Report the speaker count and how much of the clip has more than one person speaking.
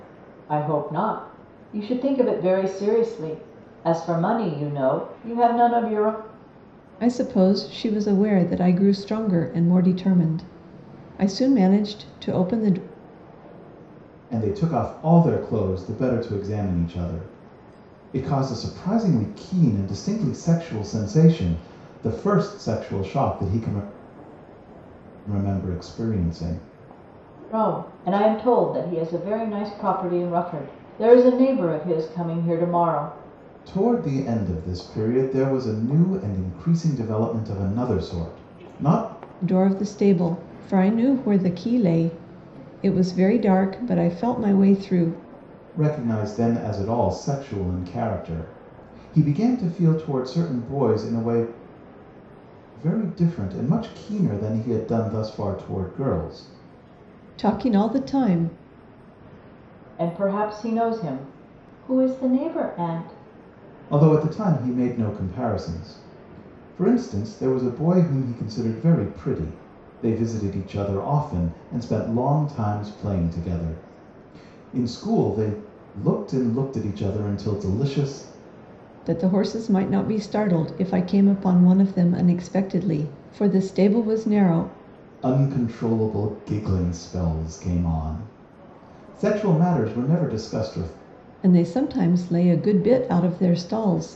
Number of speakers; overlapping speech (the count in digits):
3, no overlap